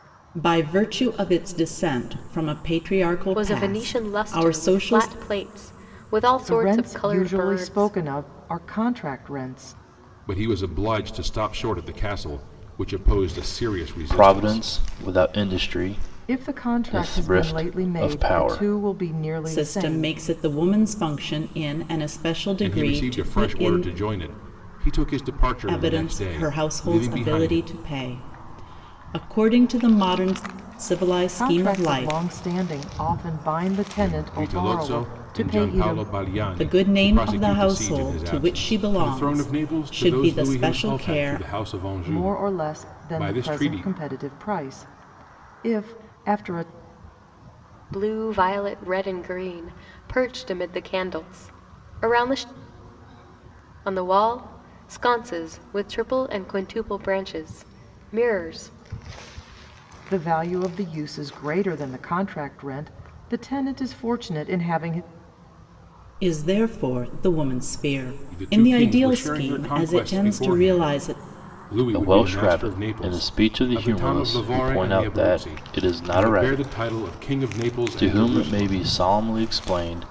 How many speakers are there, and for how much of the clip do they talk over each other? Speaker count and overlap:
five, about 35%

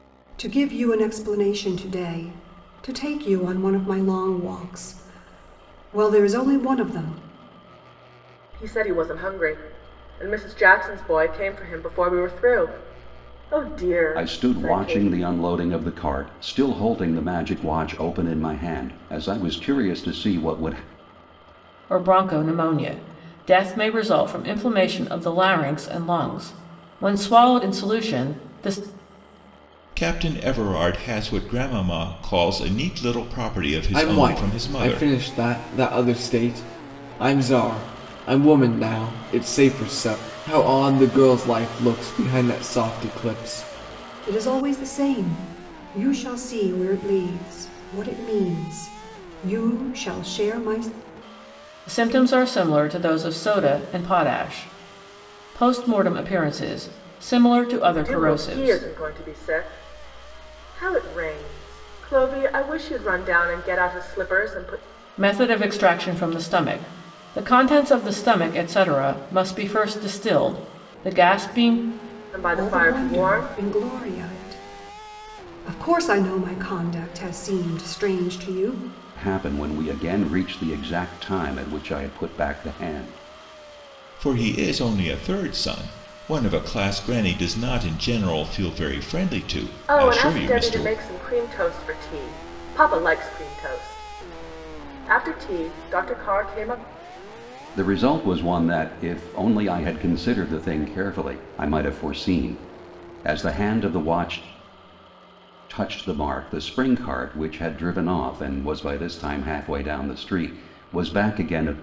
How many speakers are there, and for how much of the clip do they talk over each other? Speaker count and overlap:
six, about 5%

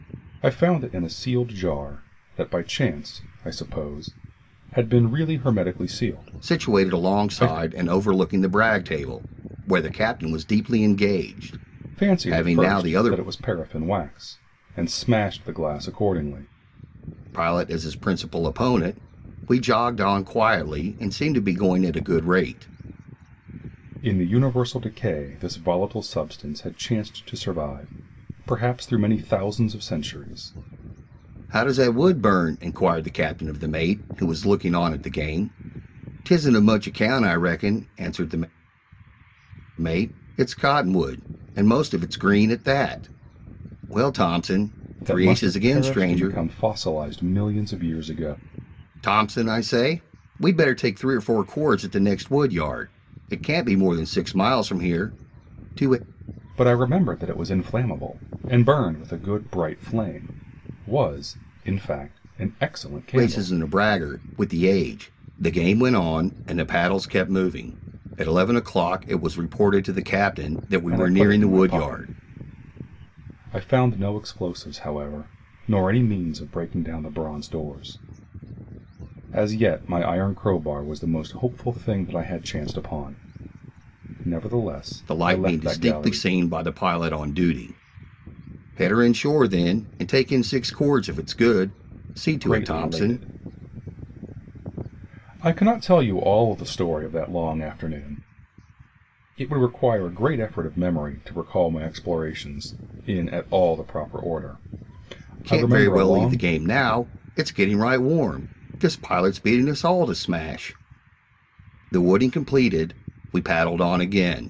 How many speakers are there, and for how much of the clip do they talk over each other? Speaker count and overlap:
two, about 8%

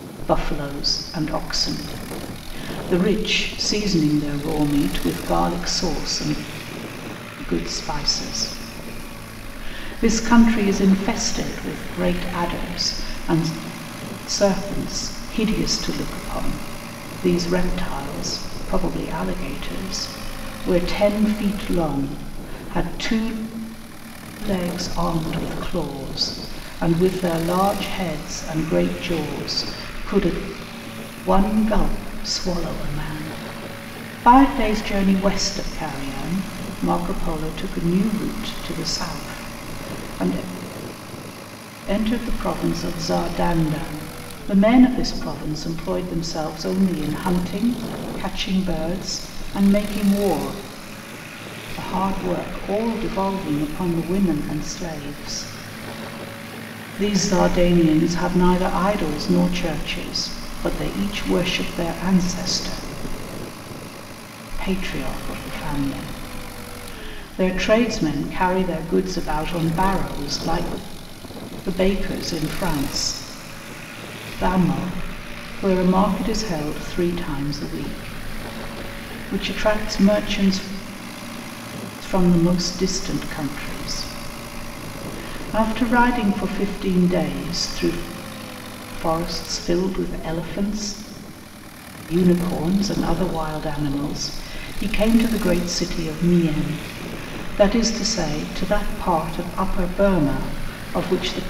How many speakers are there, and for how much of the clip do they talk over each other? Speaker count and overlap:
one, no overlap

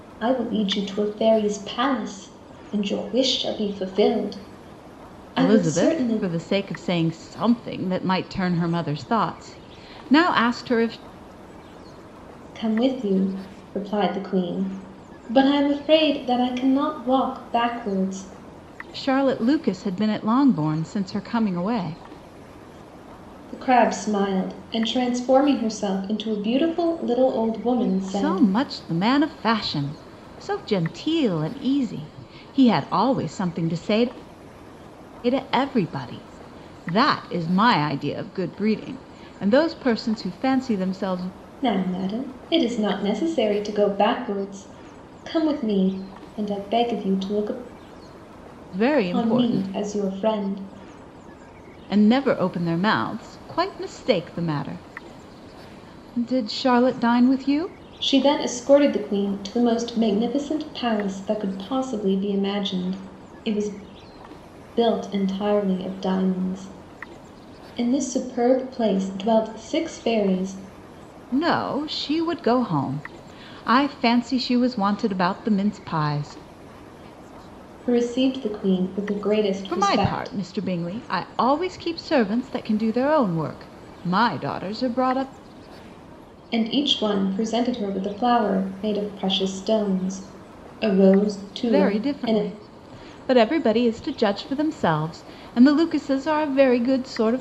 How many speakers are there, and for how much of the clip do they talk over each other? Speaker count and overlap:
two, about 4%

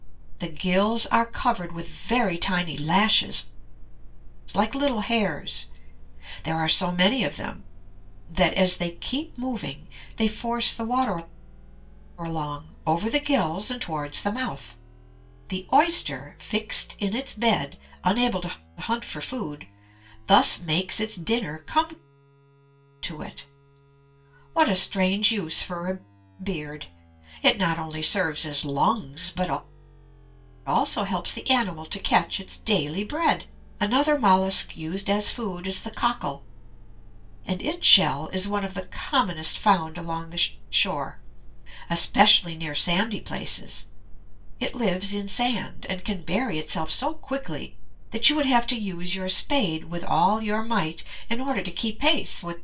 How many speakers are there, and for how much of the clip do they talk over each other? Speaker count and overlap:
one, no overlap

